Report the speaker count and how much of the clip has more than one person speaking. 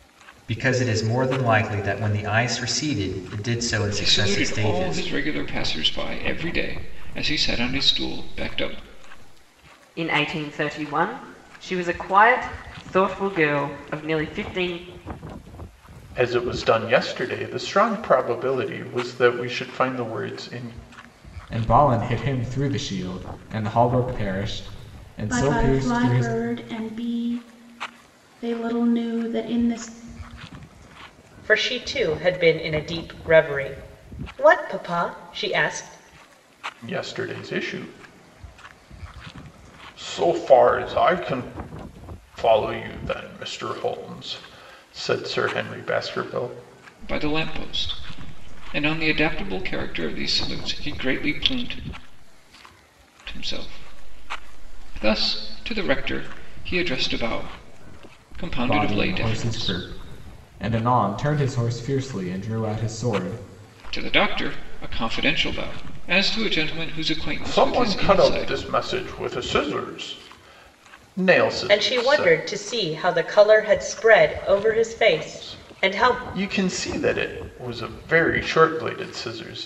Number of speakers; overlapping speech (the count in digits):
7, about 8%